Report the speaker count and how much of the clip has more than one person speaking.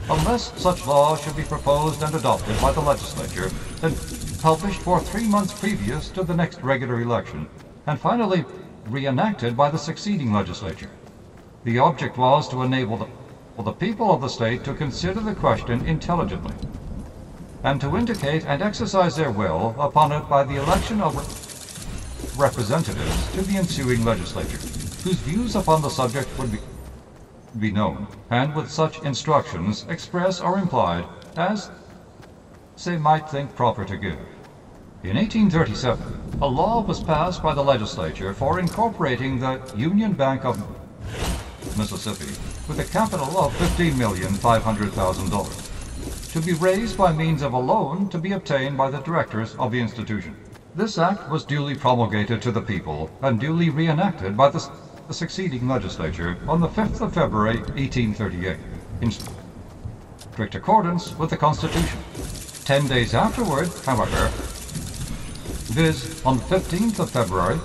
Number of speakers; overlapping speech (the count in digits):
1, no overlap